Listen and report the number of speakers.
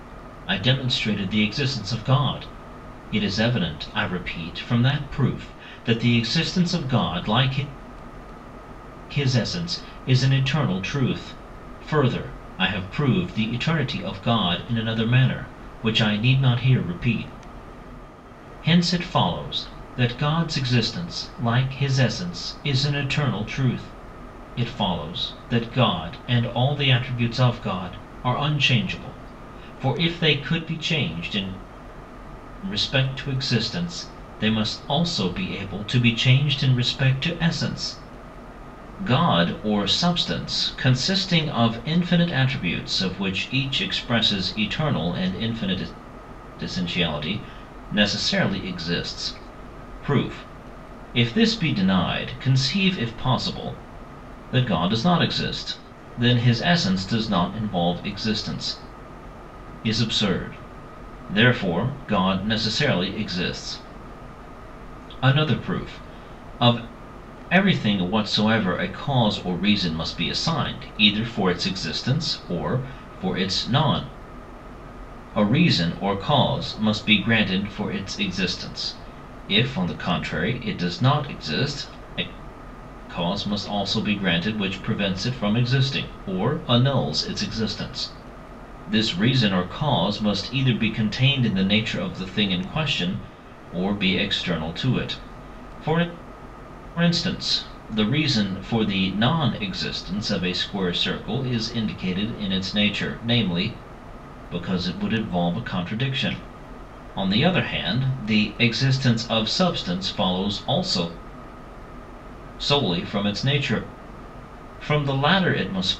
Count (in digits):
1